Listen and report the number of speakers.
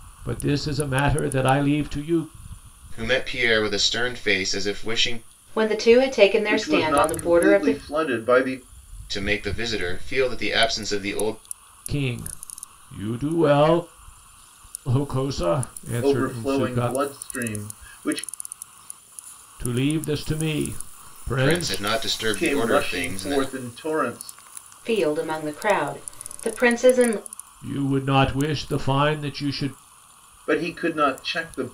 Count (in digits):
4